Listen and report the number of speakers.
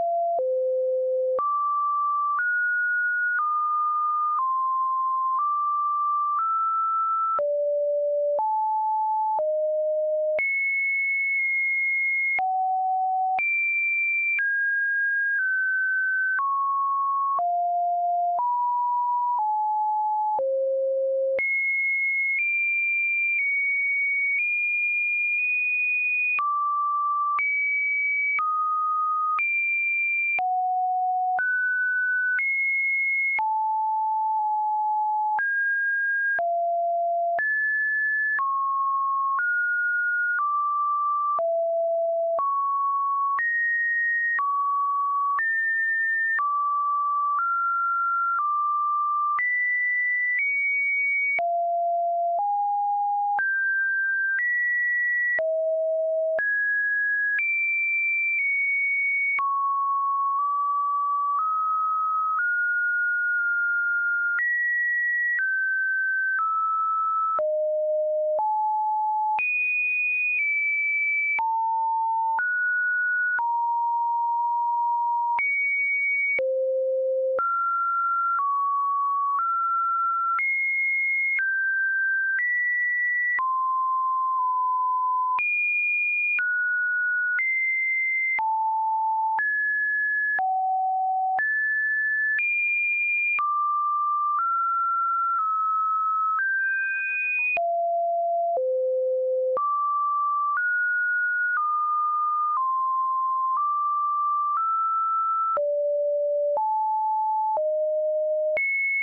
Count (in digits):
0